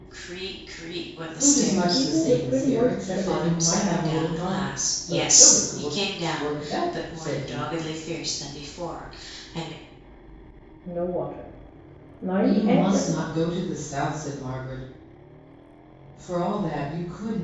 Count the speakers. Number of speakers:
3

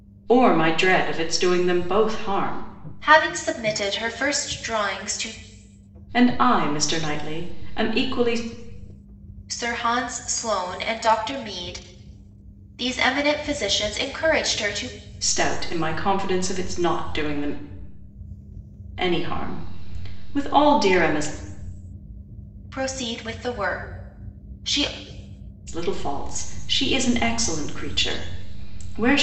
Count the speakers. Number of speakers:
2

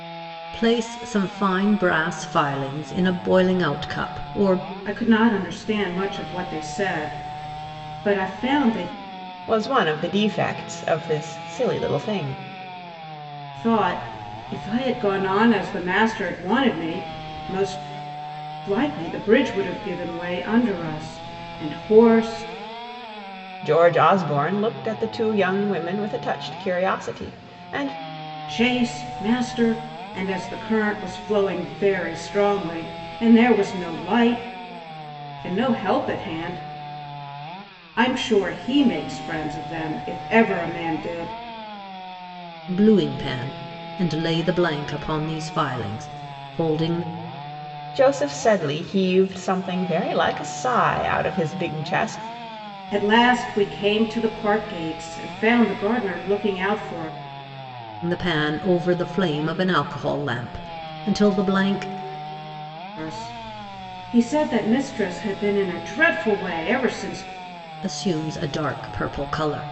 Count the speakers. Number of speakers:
3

